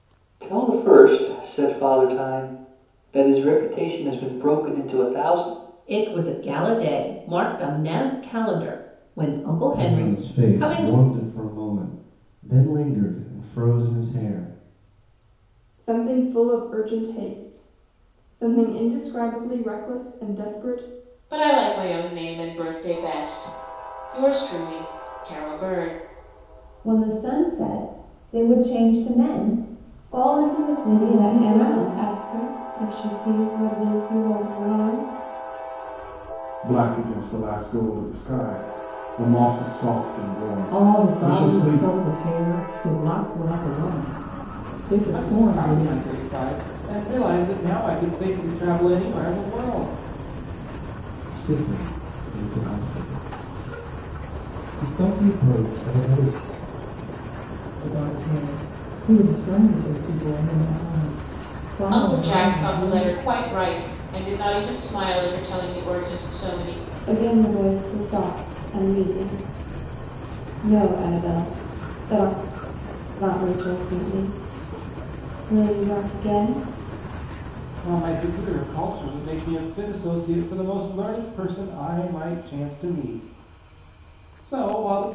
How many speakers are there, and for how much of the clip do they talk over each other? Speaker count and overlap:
10, about 7%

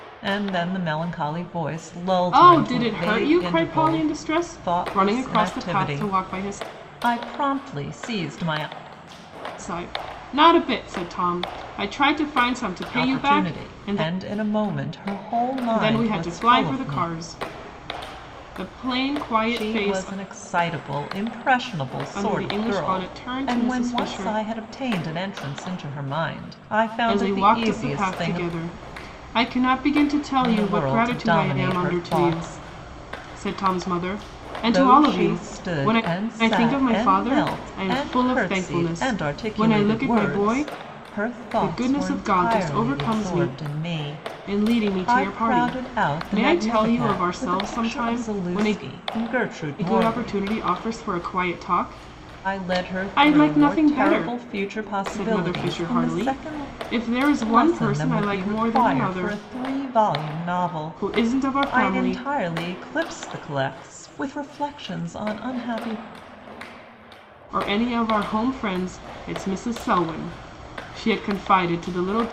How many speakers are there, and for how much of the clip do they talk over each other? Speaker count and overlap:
2, about 44%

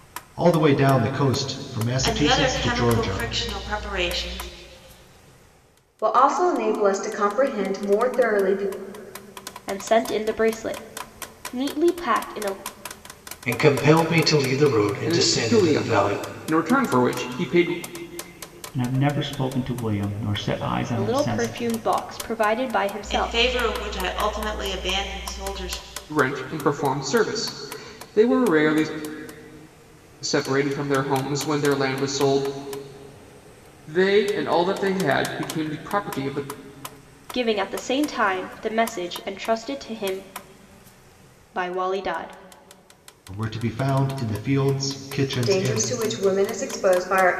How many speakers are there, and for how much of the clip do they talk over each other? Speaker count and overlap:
7, about 11%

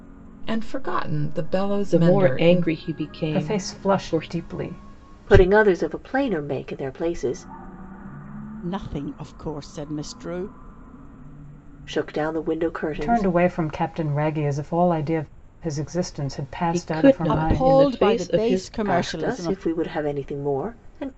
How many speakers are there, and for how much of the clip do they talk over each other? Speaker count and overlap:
5, about 26%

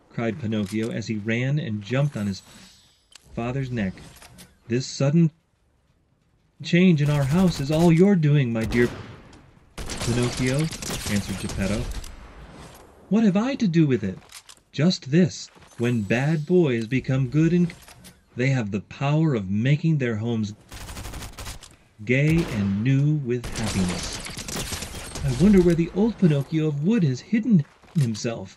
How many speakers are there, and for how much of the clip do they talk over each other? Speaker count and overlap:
1, no overlap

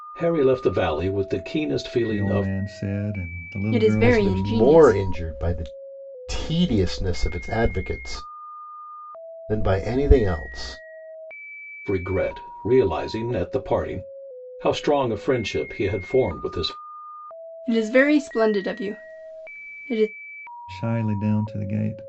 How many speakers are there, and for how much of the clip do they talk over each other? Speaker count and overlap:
4, about 8%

